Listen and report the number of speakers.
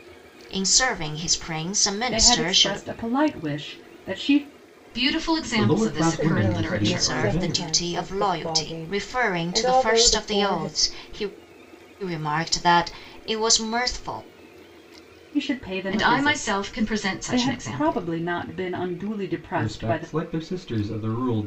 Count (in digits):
5